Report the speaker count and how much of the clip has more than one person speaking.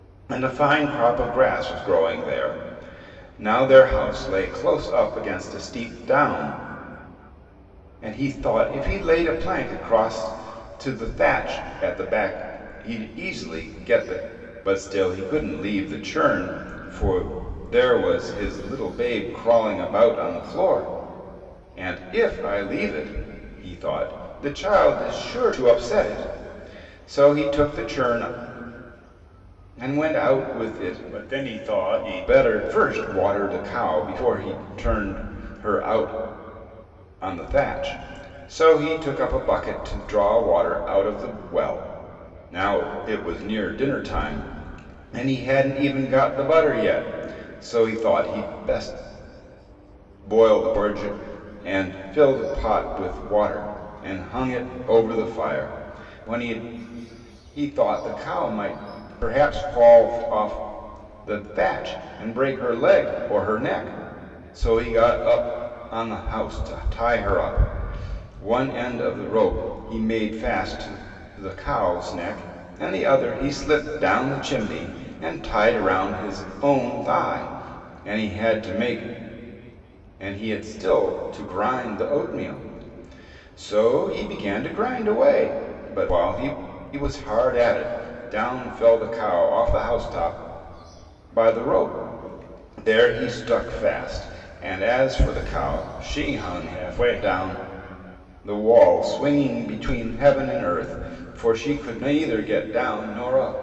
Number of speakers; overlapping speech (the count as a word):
one, no overlap